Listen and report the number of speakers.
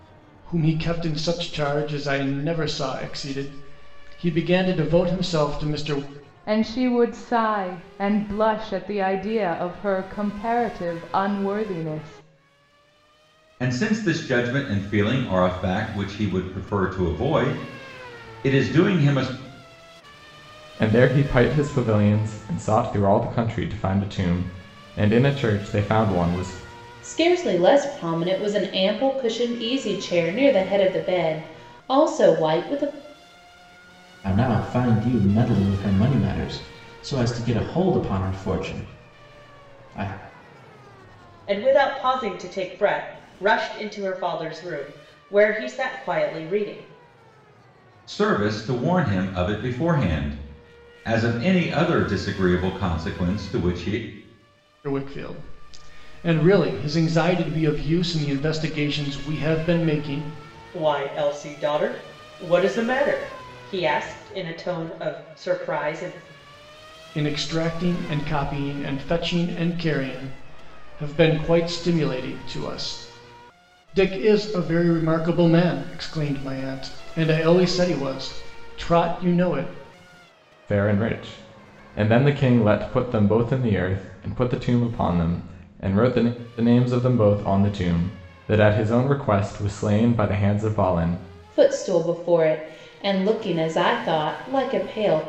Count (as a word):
seven